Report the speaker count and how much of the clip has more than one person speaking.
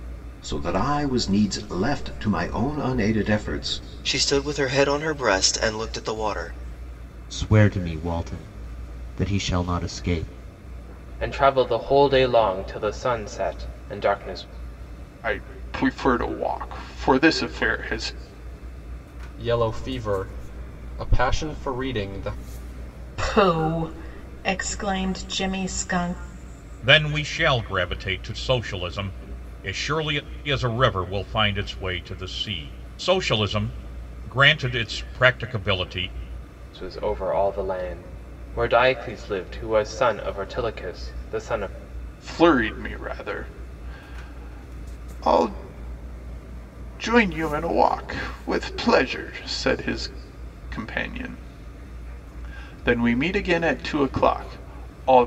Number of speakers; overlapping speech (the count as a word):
eight, no overlap